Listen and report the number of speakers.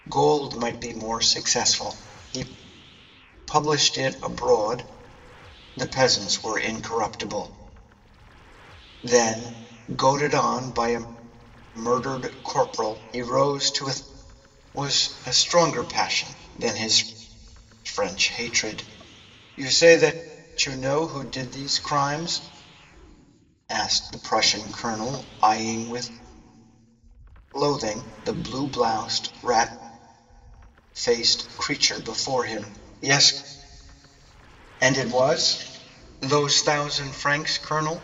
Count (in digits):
1